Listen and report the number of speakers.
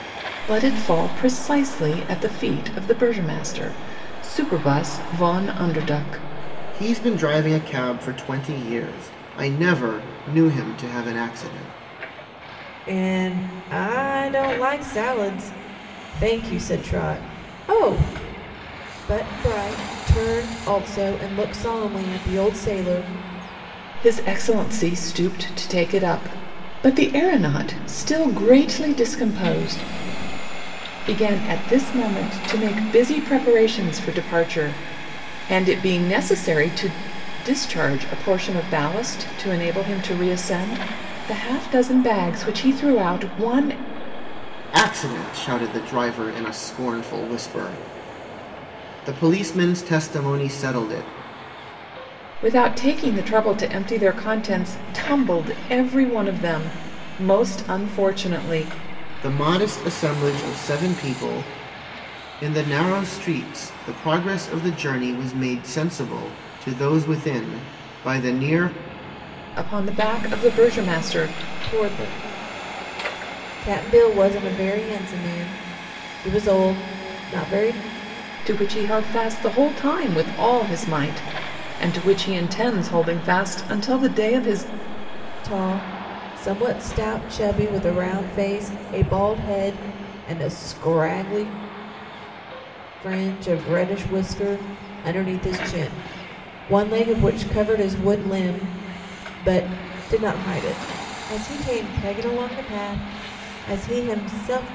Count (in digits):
3